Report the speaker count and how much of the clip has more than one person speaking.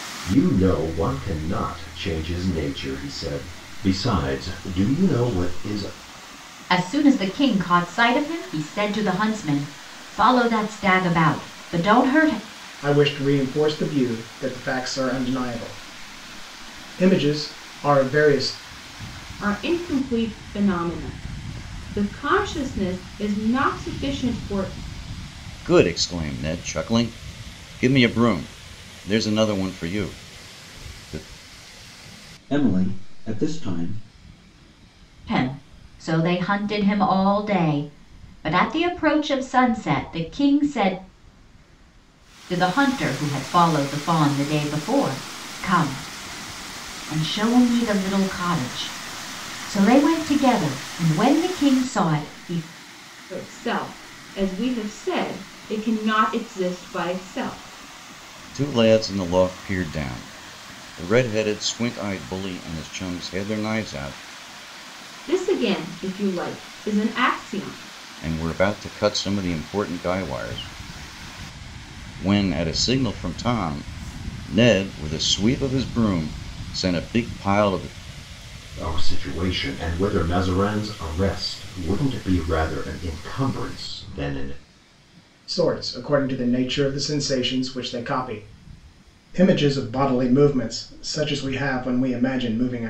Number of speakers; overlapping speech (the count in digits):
6, no overlap